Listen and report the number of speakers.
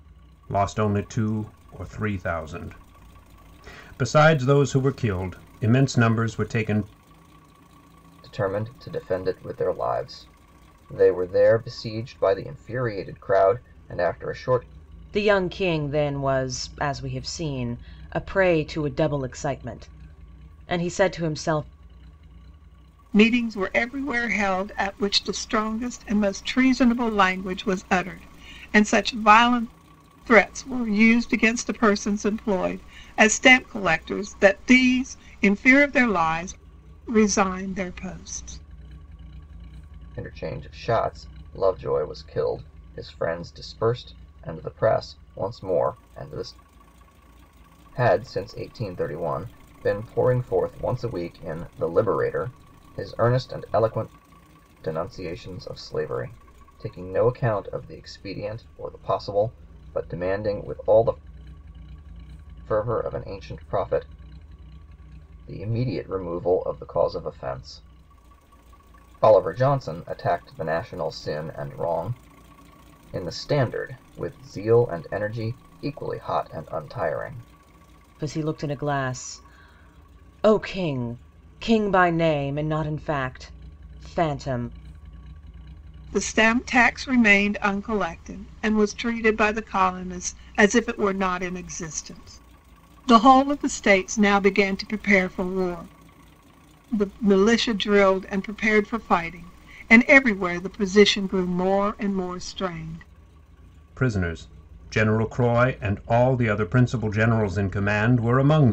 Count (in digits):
4